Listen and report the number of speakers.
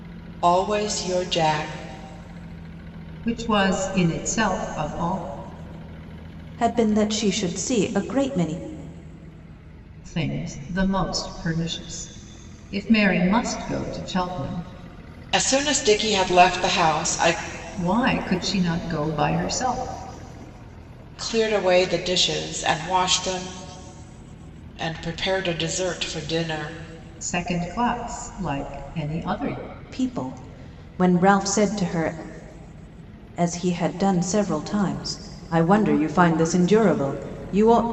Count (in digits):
3